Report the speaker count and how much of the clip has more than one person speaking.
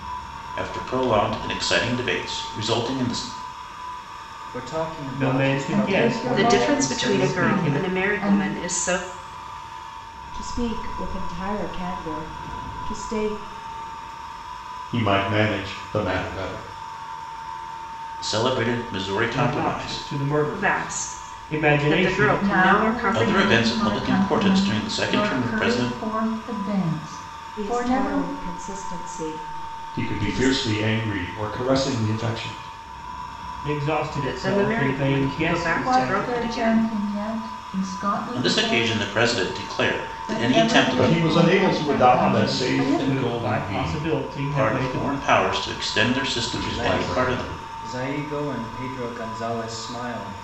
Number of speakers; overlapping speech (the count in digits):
7, about 39%